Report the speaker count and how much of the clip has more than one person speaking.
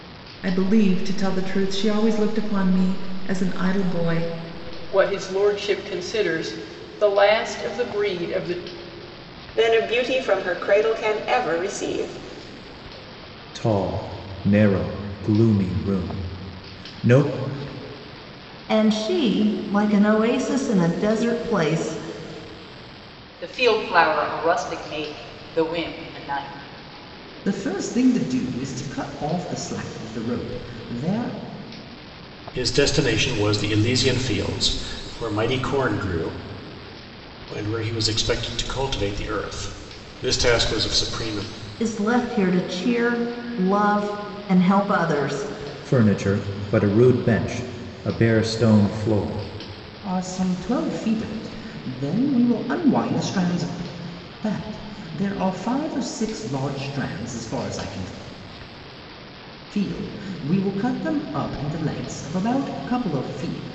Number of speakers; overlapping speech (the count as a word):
eight, no overlap